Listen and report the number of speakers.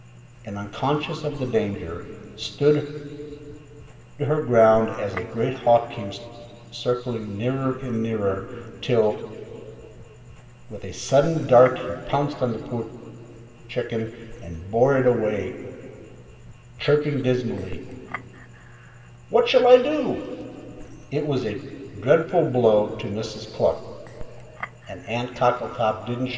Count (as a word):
one